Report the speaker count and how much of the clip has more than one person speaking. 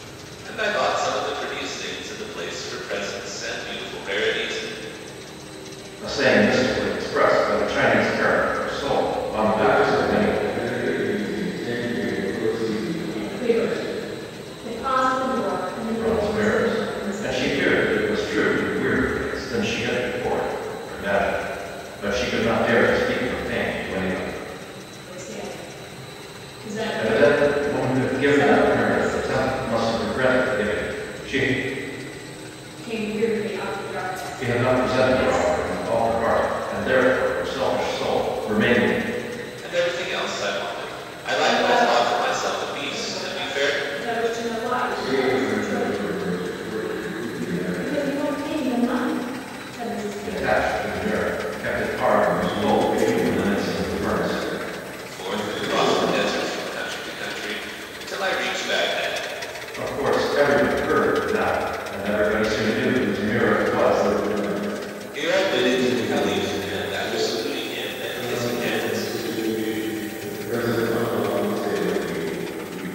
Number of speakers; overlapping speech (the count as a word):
four, about 28%